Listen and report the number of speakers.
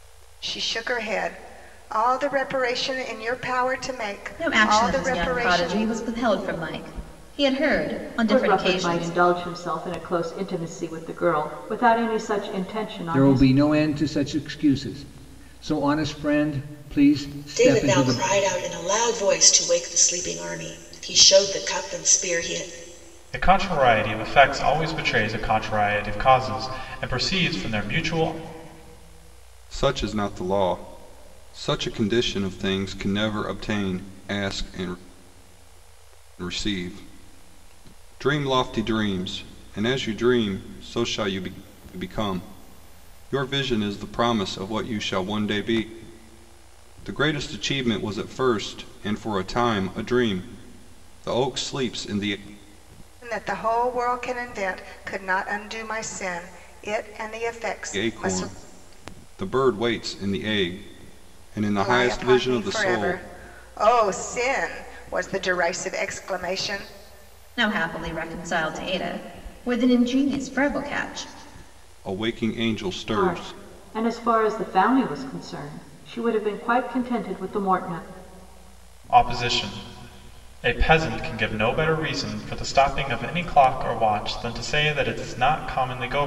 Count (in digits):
7